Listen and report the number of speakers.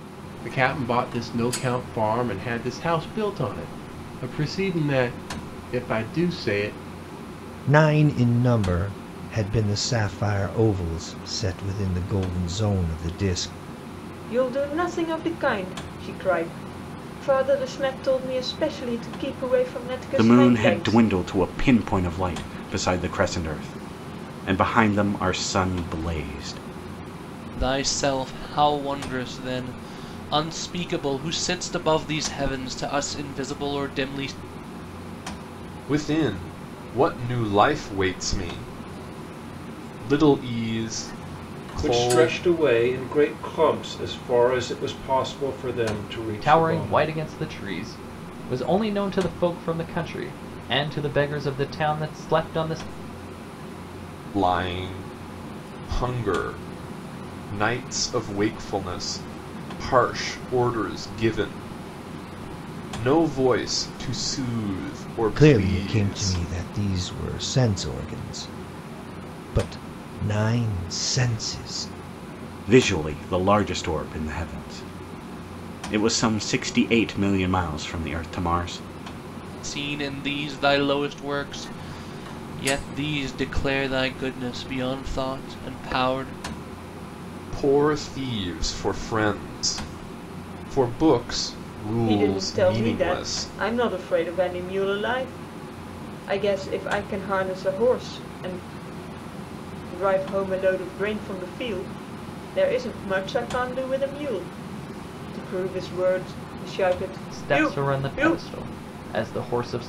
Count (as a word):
eight